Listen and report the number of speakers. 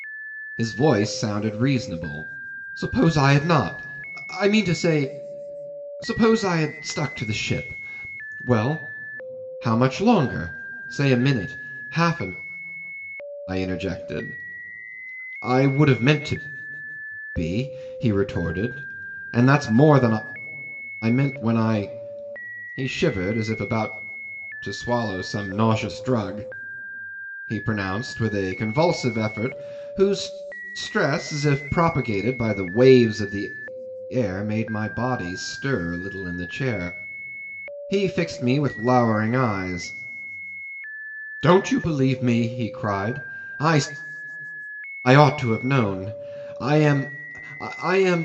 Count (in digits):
1